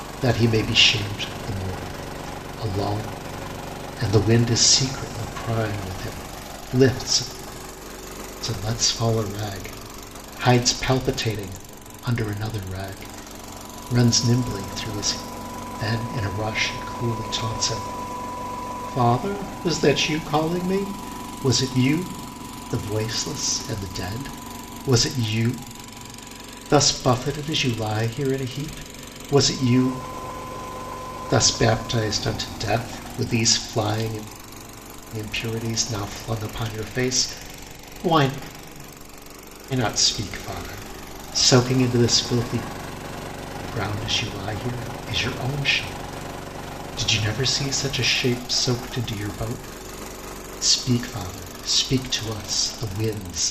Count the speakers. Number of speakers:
one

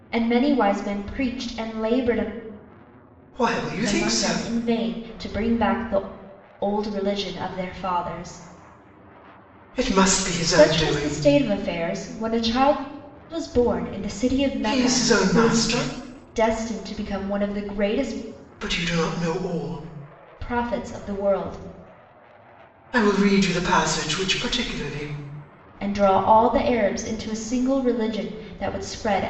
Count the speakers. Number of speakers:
two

